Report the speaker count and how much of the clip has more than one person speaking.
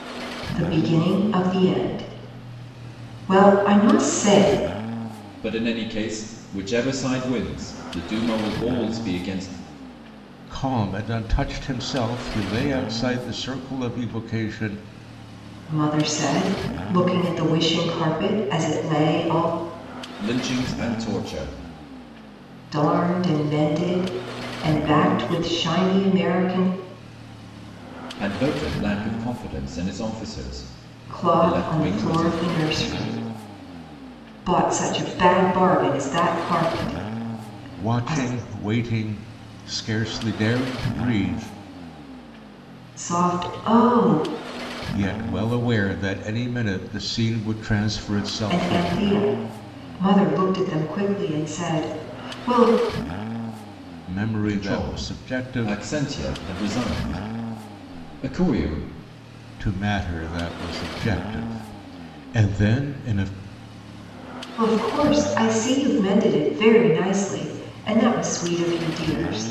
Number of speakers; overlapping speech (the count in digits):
3, about 5%